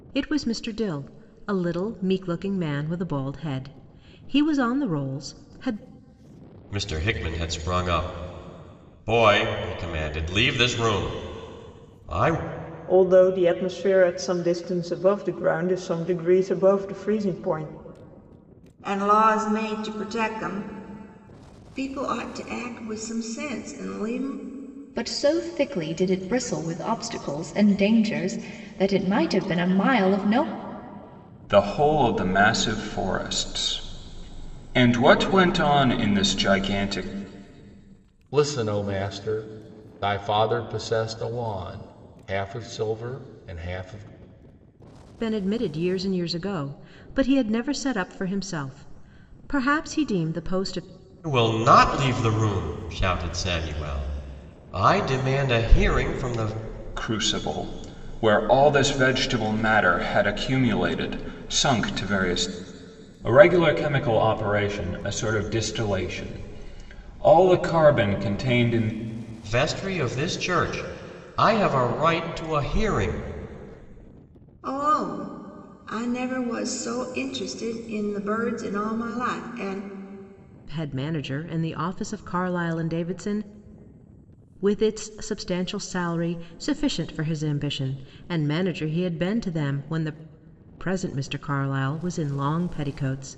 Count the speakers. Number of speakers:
7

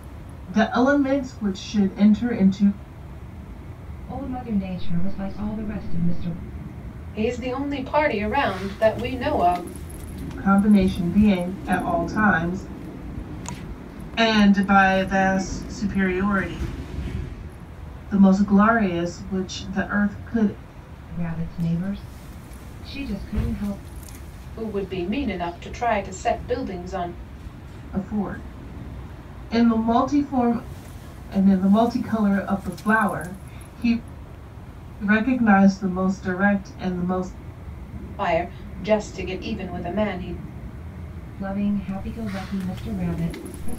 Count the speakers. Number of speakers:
3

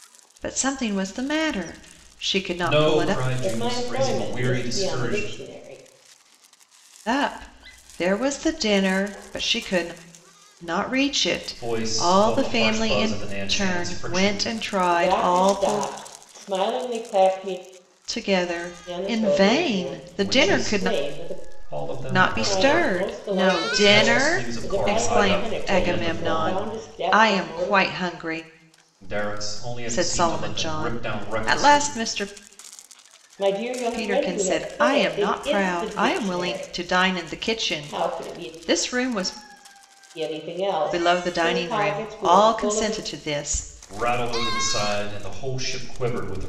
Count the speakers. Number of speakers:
3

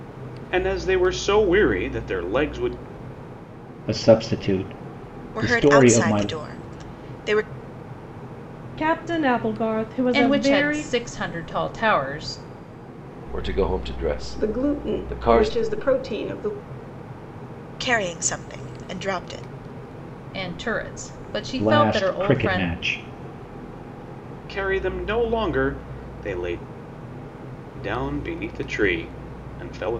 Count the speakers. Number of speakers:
7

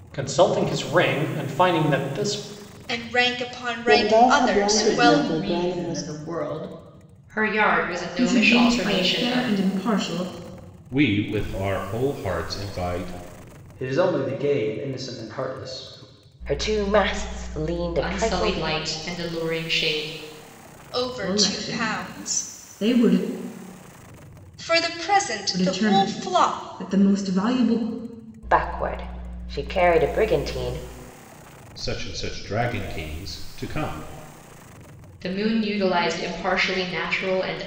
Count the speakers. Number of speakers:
9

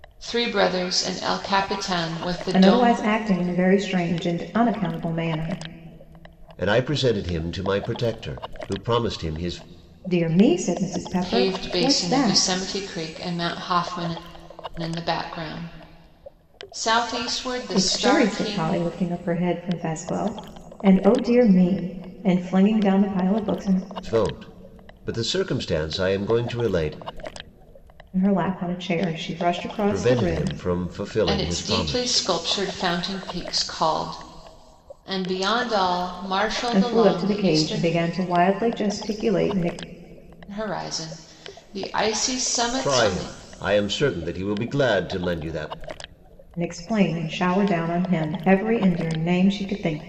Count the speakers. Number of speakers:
3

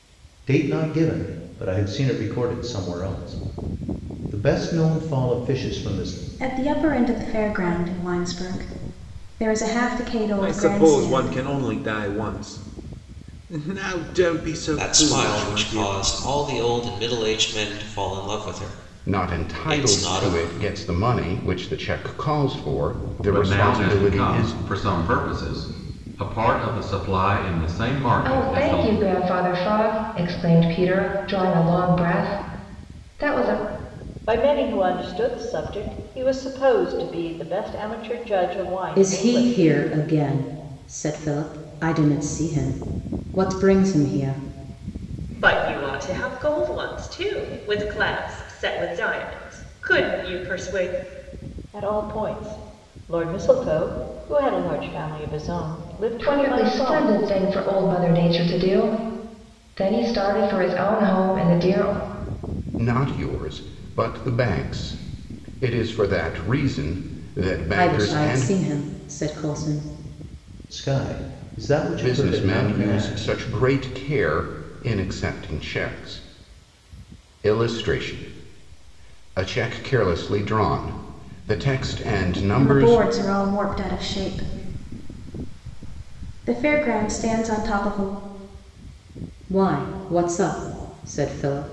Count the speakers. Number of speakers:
10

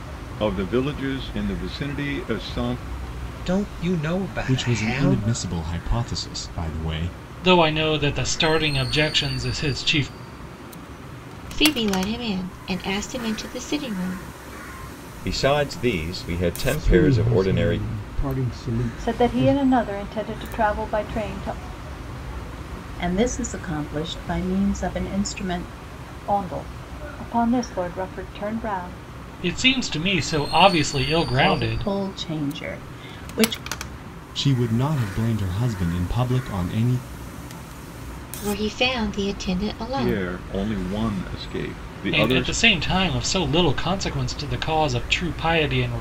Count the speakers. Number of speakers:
9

